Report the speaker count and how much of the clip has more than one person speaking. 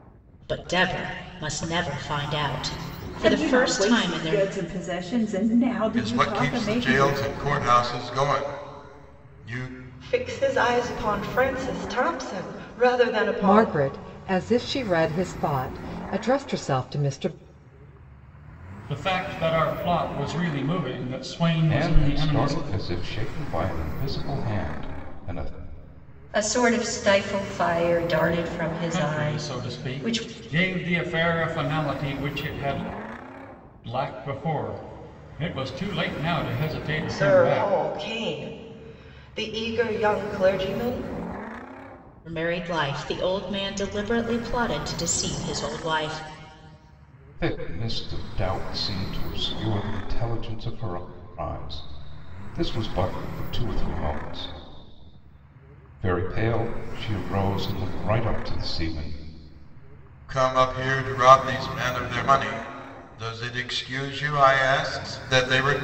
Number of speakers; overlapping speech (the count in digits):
8, about 9%